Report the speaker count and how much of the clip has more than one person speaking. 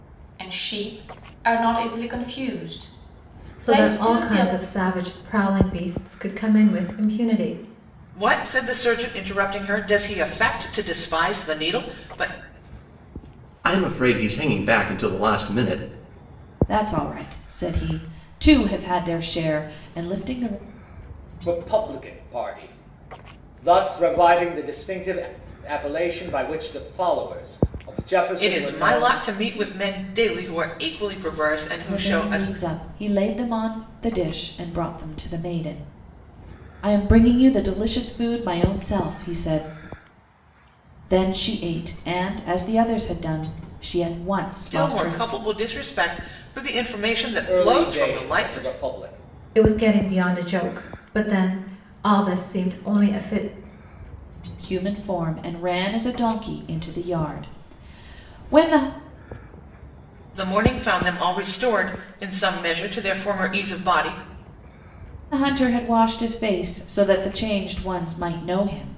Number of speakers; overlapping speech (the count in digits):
6, about 7%